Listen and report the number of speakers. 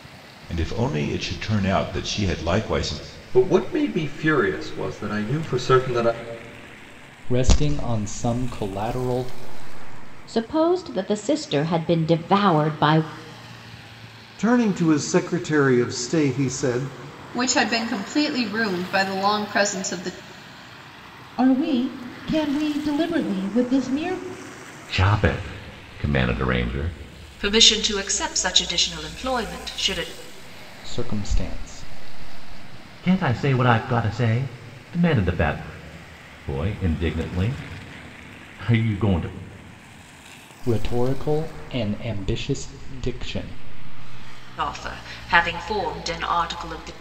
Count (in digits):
9